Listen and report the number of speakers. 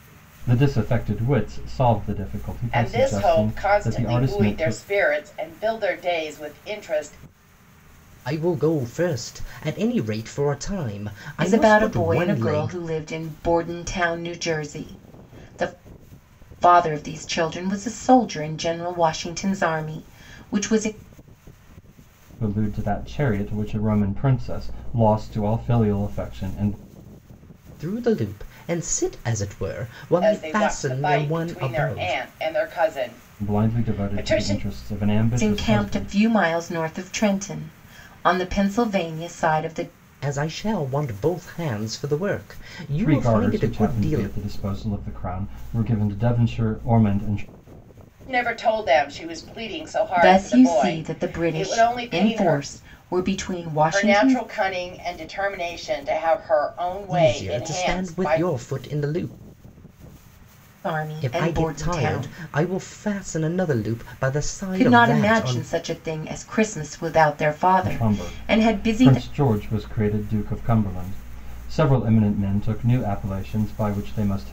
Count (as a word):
four